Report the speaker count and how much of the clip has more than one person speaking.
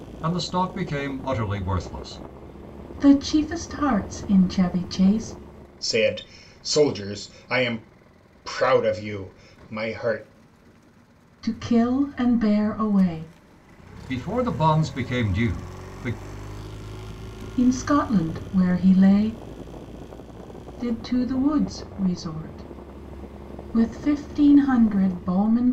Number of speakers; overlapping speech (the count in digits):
3, no overlap